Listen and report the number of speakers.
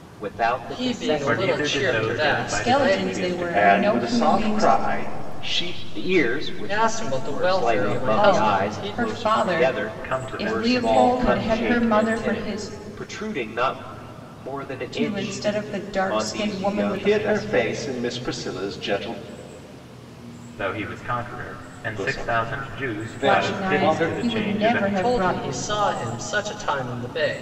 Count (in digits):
6